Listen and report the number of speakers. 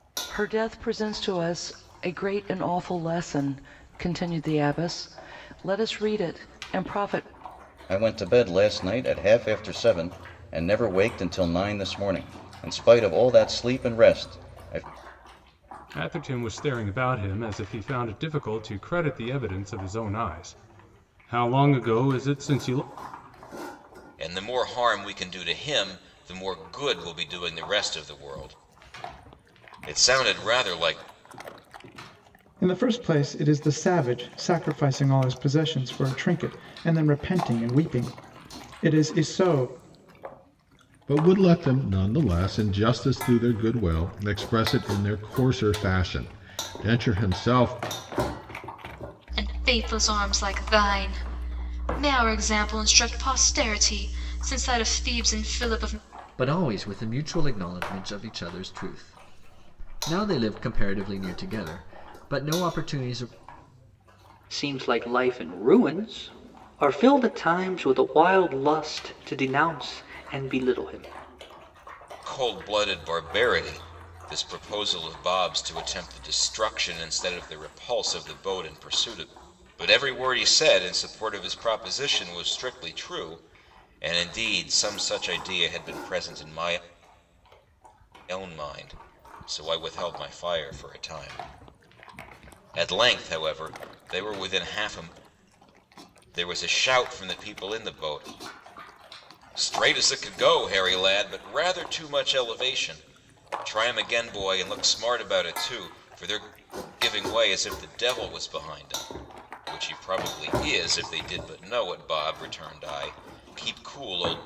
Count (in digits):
9